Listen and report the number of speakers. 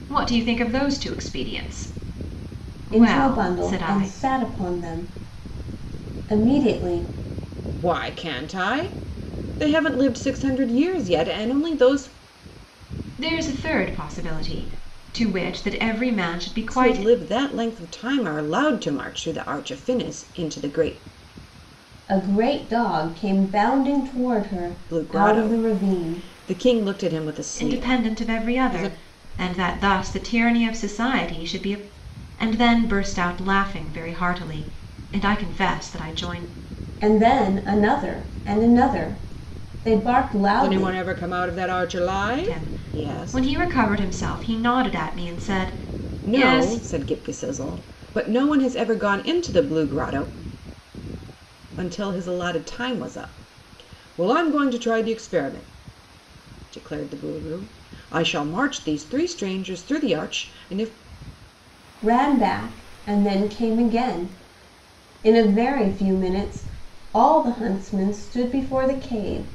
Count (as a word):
three